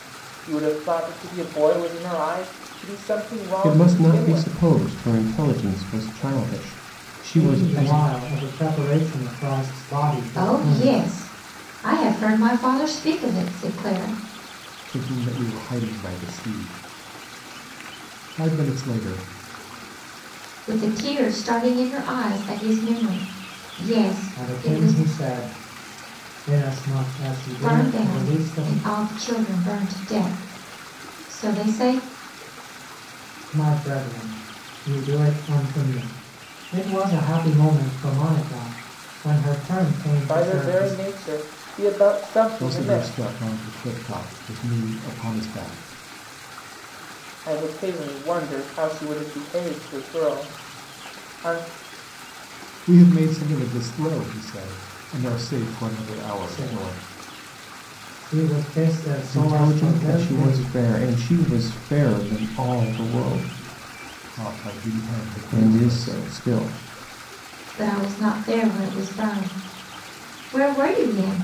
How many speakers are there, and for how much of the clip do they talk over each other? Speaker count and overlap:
five, about 12%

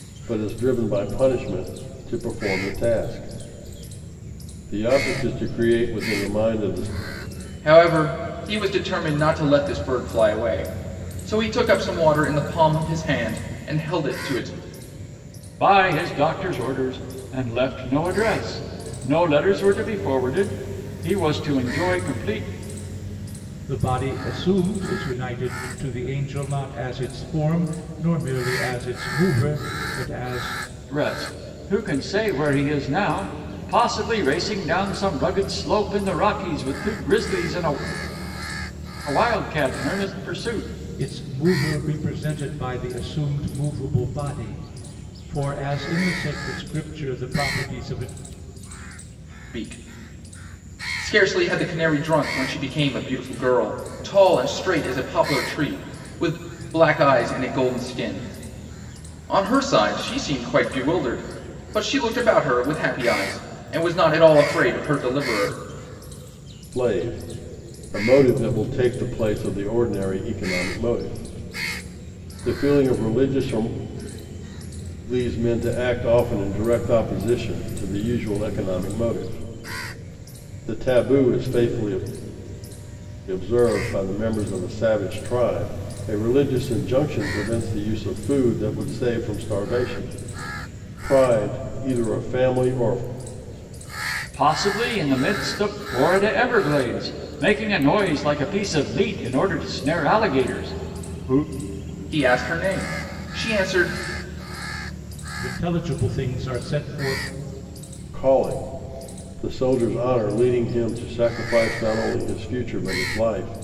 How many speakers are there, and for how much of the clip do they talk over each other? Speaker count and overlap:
four, no overlap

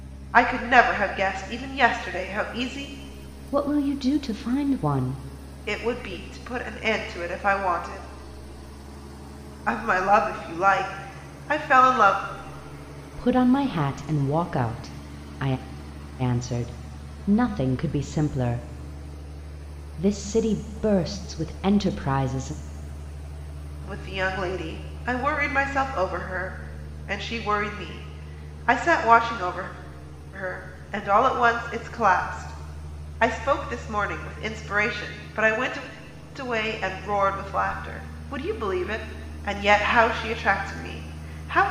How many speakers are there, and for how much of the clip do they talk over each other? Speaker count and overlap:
two, no overlap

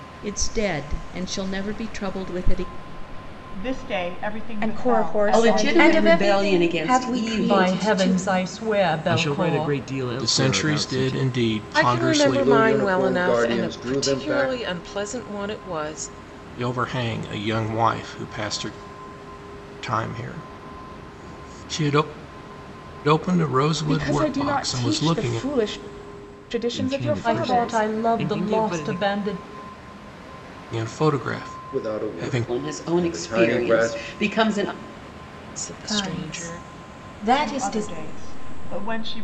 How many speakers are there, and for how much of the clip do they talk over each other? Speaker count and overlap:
ten, about 41%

